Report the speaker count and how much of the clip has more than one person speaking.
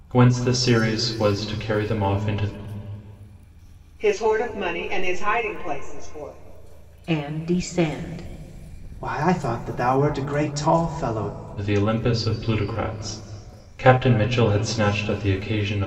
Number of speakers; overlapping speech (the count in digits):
4, no overlap